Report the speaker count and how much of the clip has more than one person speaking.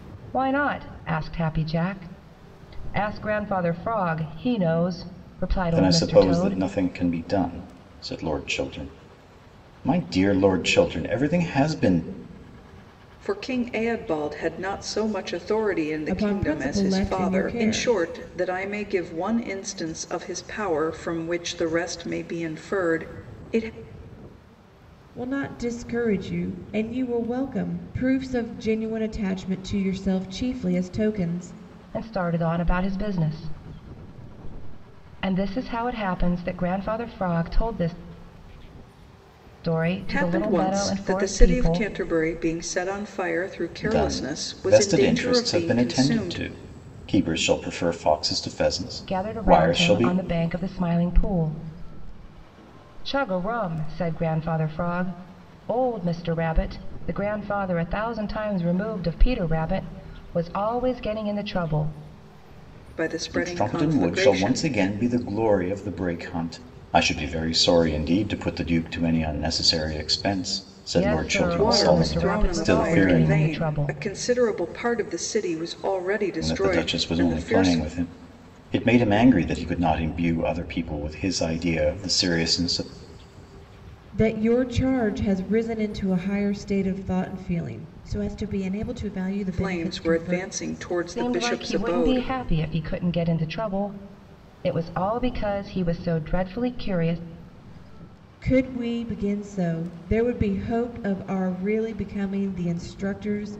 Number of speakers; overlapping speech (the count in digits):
4, about 16%